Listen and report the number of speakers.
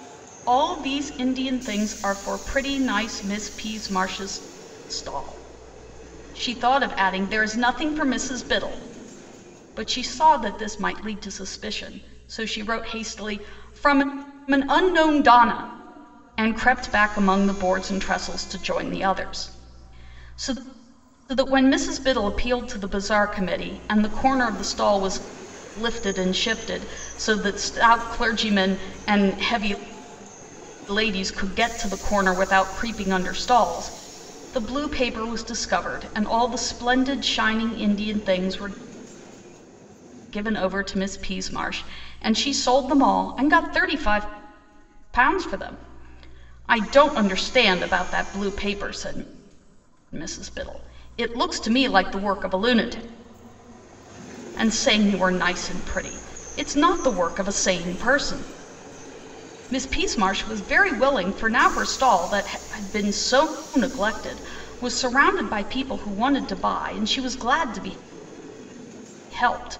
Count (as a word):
one